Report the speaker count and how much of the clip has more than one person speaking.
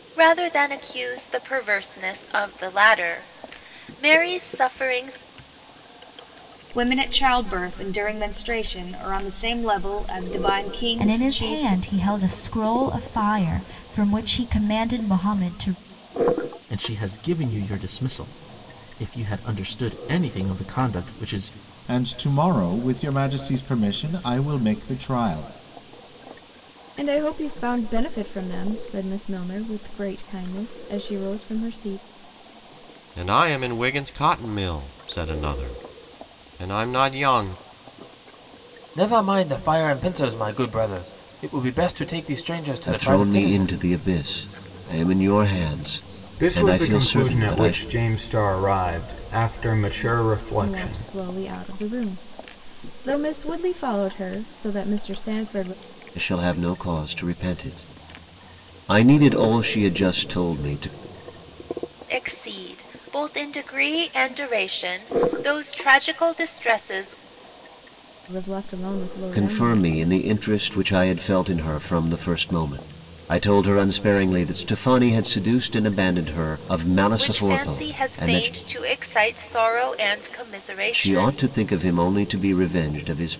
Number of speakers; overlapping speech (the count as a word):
ten, about 8%